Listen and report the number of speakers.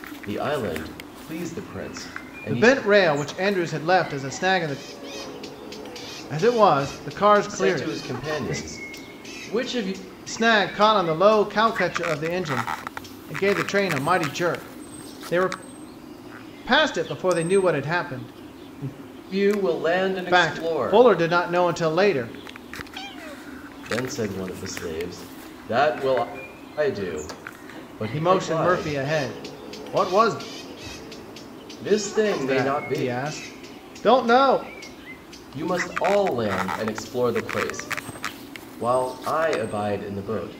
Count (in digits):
2